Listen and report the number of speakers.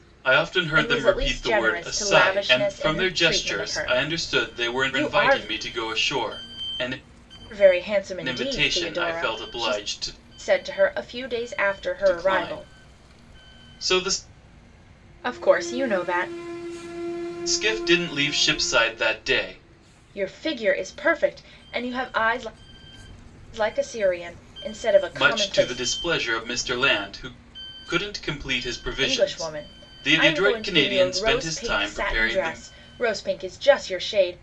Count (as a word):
two